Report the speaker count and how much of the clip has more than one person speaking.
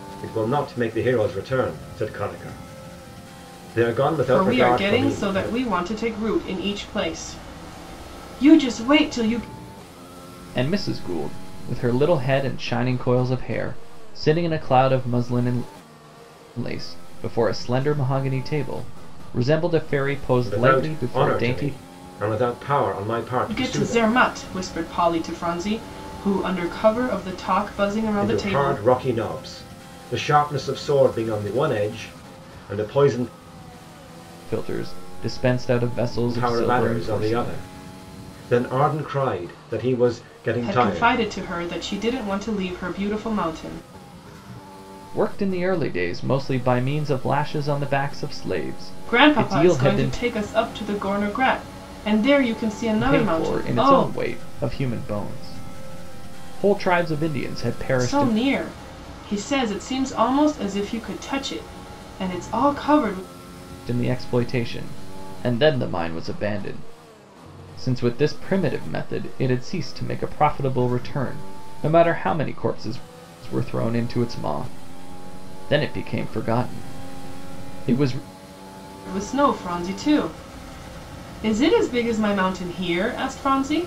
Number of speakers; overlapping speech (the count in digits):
3, about 10%